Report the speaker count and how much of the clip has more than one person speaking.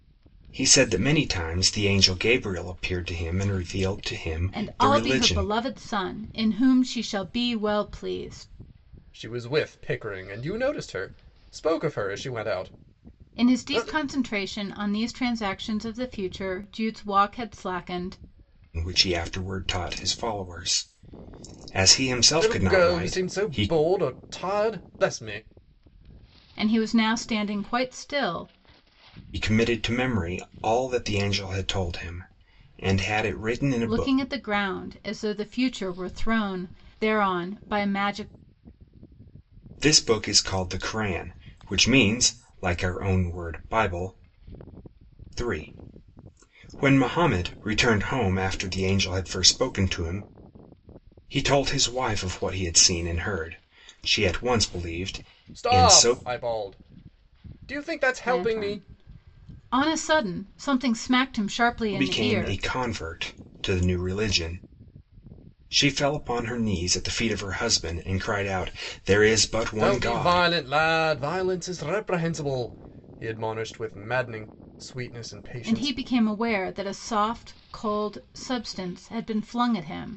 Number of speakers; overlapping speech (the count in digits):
3, about 8%